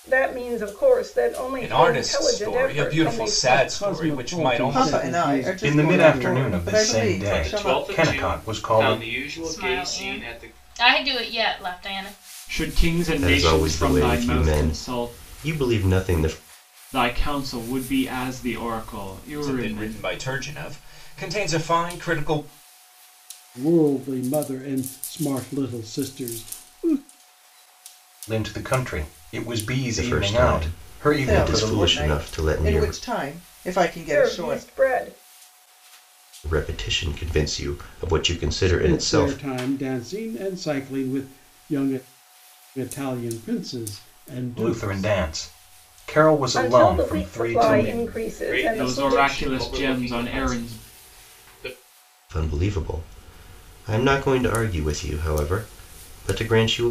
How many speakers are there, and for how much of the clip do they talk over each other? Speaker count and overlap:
nine, about 36%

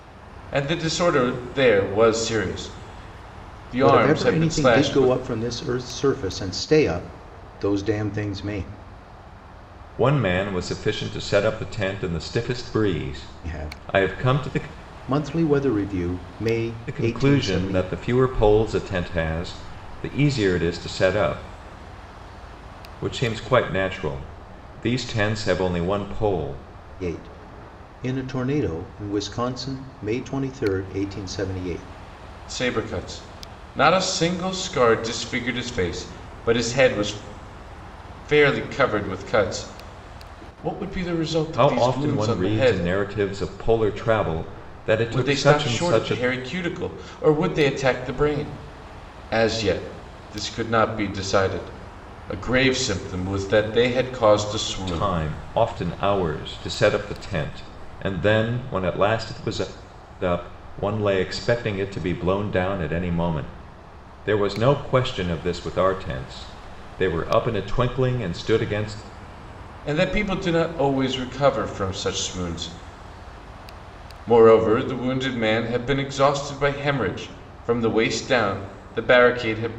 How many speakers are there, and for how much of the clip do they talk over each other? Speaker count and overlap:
three, about 8%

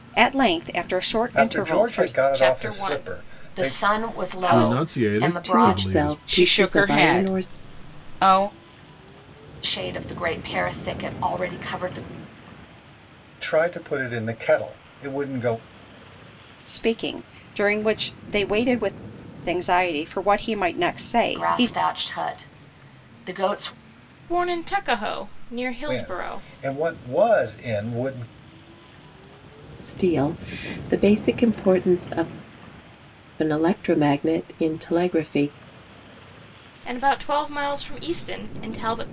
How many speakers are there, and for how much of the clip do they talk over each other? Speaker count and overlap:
seven, about 18%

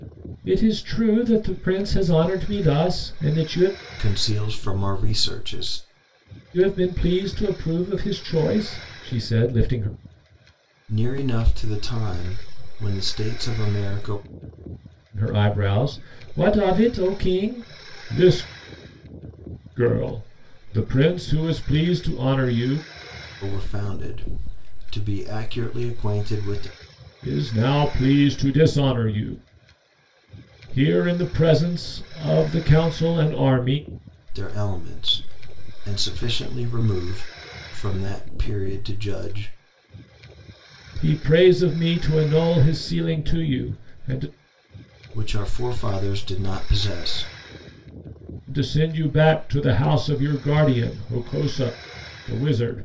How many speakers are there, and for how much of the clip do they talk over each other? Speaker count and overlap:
two, no overlap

